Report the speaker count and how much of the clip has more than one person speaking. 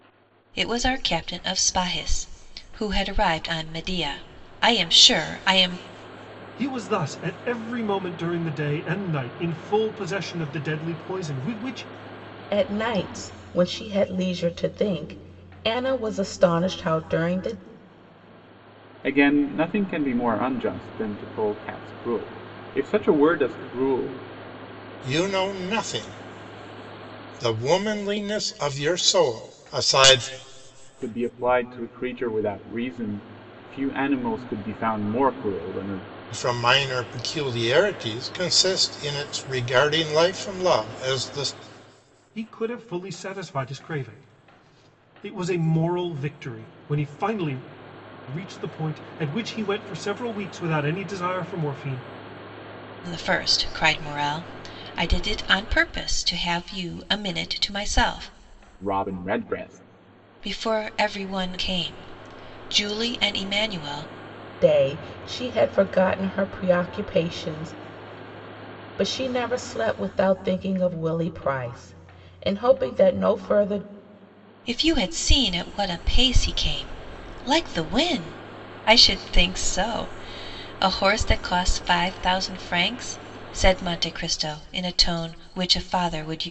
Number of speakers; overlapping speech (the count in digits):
5, no overlap